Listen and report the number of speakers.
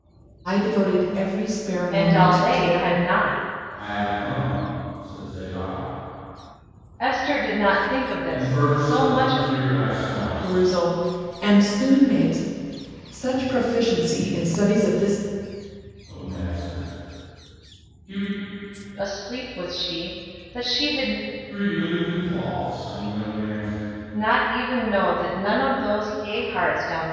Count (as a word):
three